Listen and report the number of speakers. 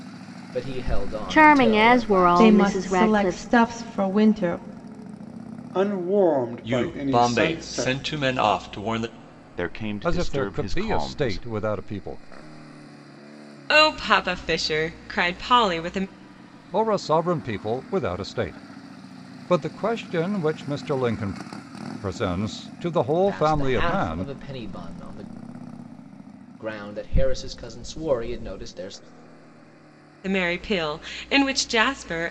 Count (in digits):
8